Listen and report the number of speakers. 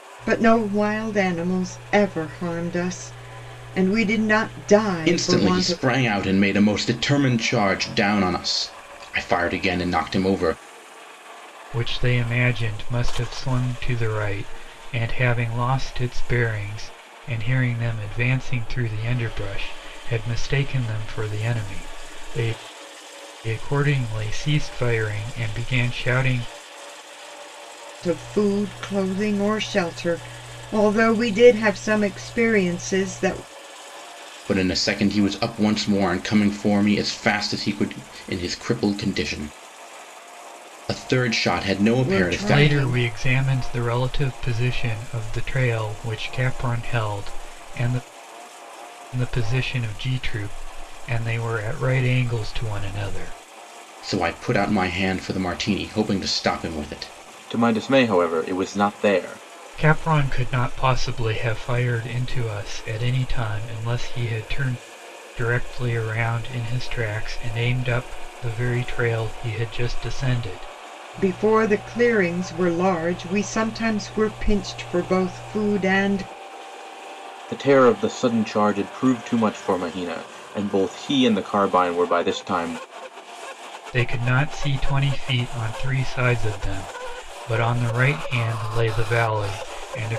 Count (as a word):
three